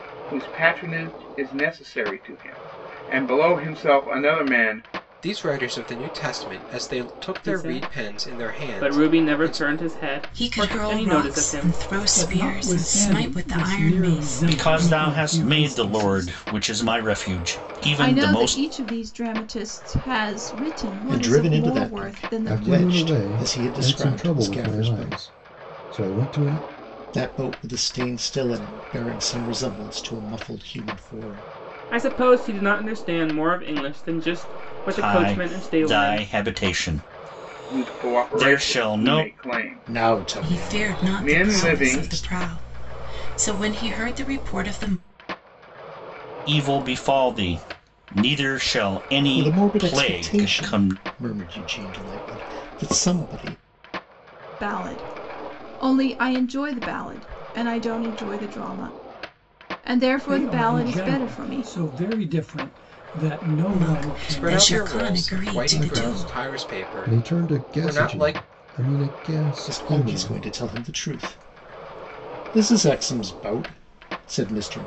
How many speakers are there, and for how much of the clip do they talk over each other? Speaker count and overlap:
9, about 36%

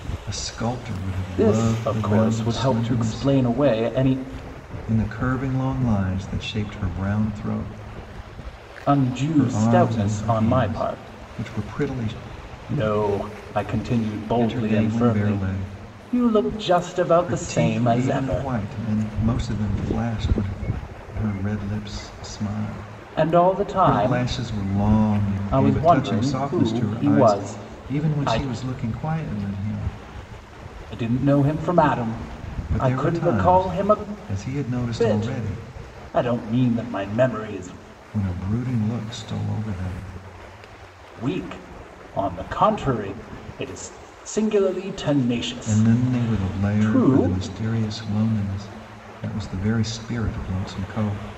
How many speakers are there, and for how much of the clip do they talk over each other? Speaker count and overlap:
2, about 30%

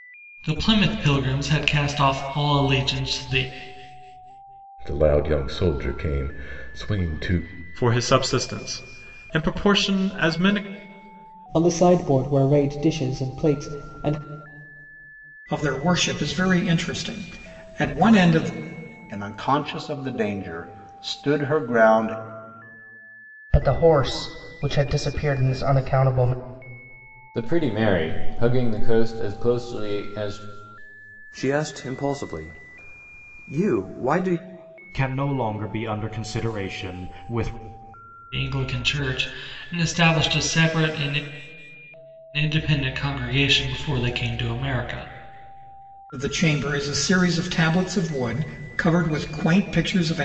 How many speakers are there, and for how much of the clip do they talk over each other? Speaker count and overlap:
10, no overlap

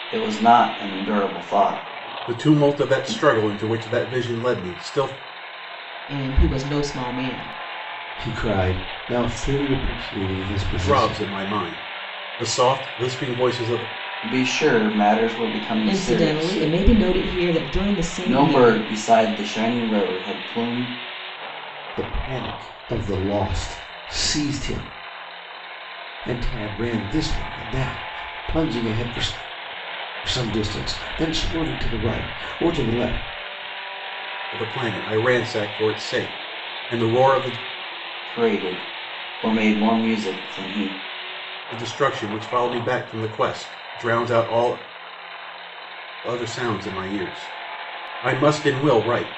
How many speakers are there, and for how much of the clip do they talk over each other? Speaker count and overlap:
4, about 6%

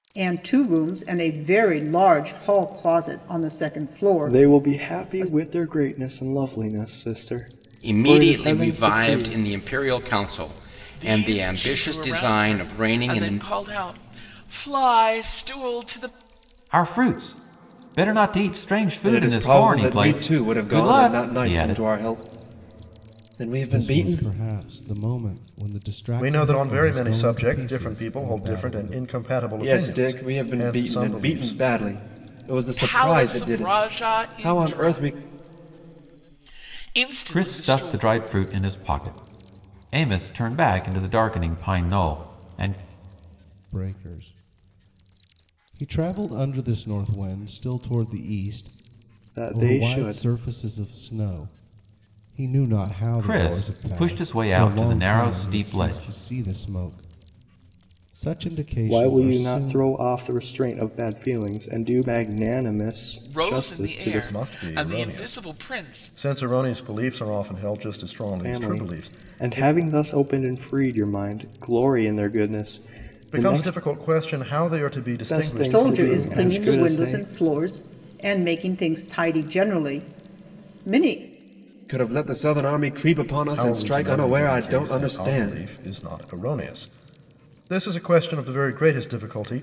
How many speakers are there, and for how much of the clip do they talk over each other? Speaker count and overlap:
8, about 34%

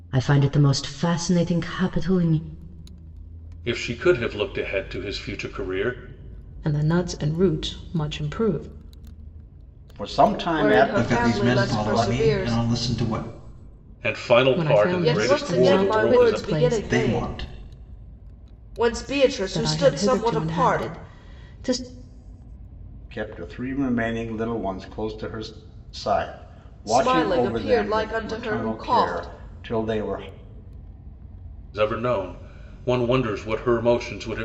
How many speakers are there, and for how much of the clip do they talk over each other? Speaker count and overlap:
6, about 26%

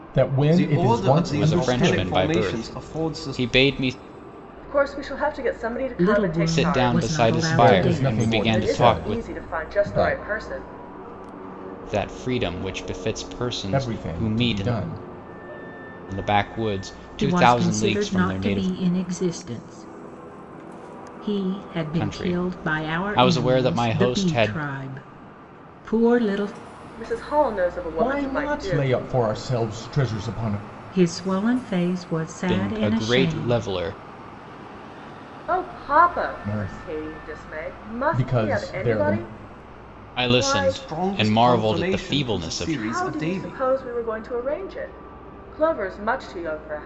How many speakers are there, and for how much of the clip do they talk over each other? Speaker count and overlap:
5, about 45%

